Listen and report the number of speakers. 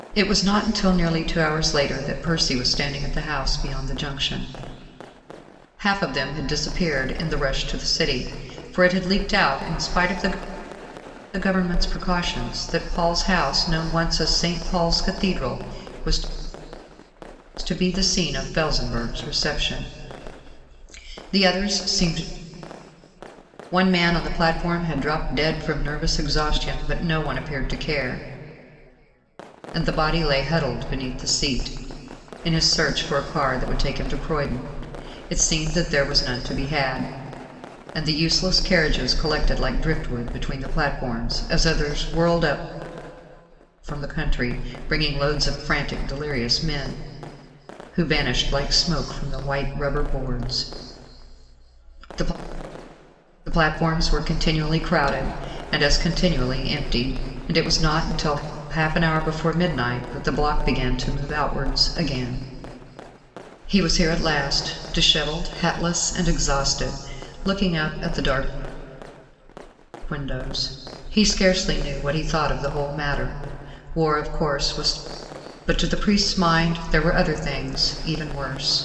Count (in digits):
1